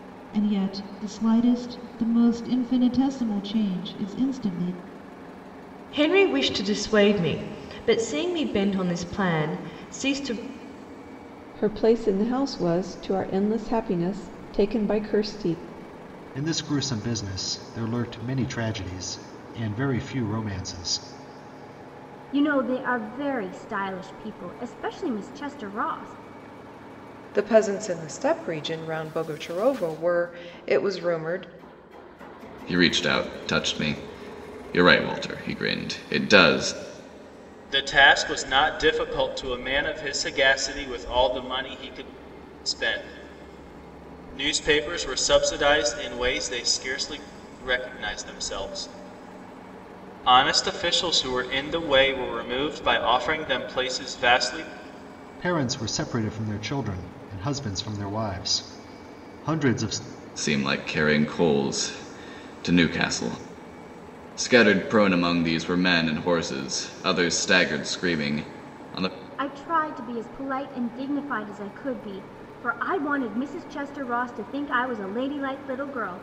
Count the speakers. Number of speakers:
8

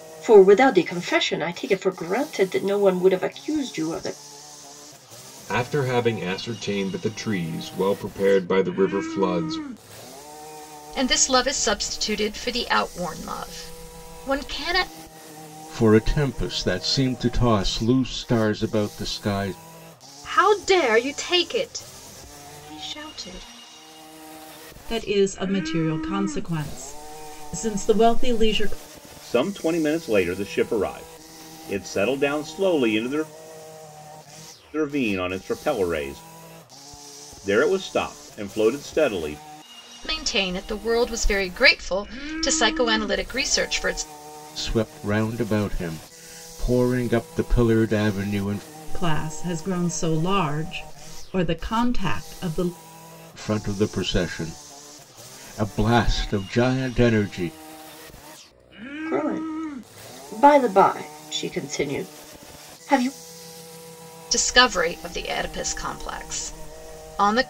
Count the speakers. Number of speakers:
7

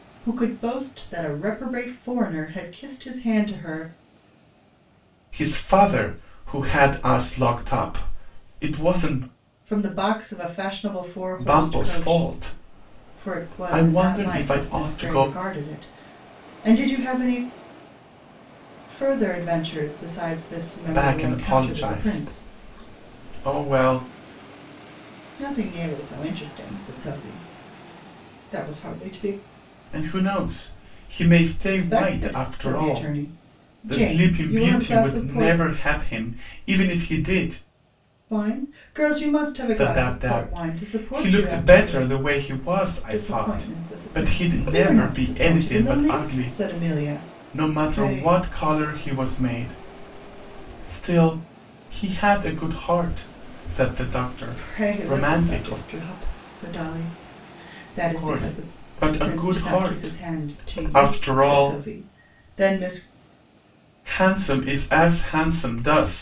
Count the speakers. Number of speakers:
2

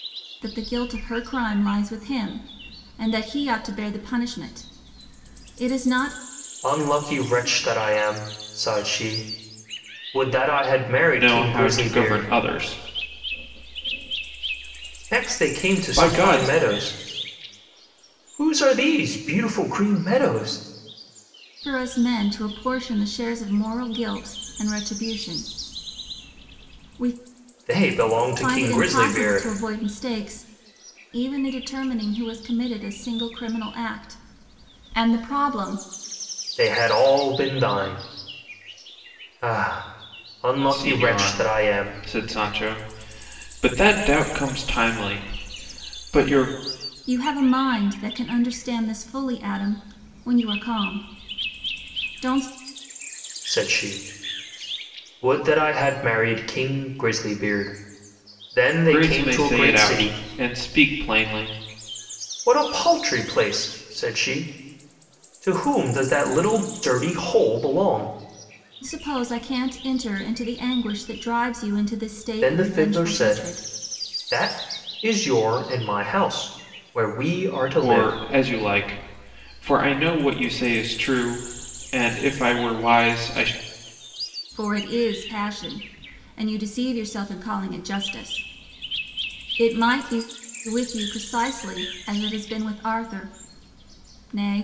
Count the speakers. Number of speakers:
3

